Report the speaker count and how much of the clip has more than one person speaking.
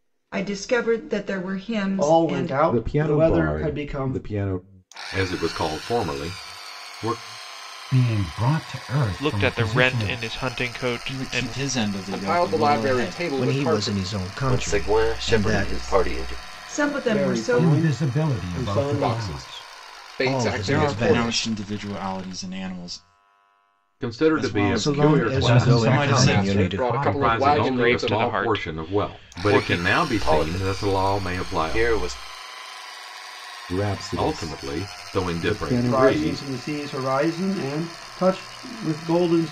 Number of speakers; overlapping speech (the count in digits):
10, about 54%